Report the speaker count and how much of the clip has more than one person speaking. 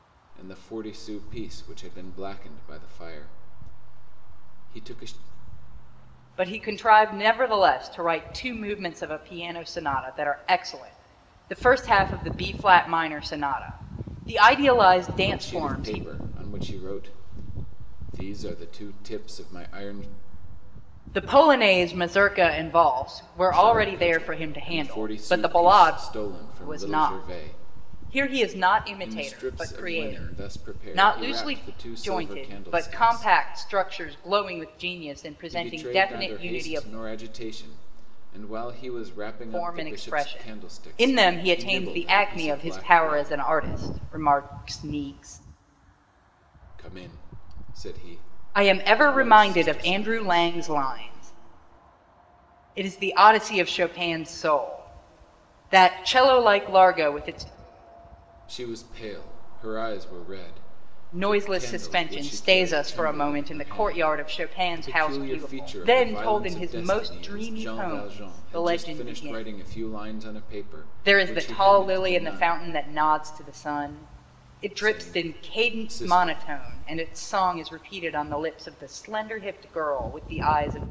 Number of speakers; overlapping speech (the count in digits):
2, about 33%